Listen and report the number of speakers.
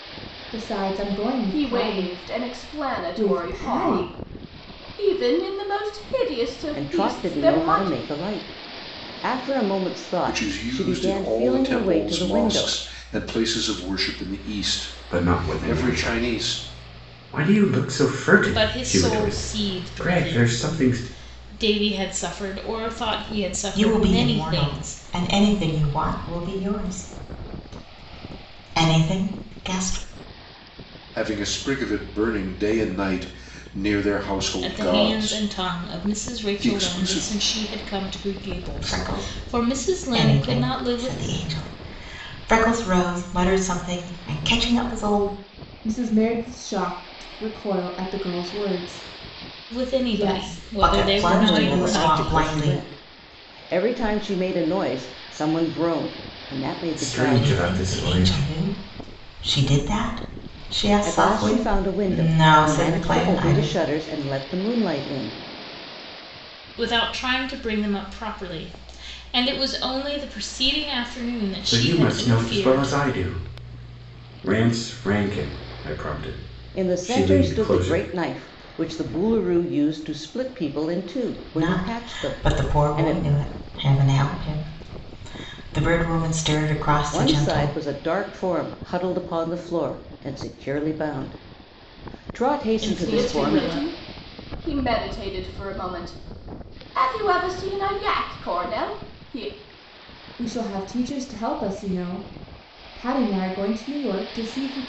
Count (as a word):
seven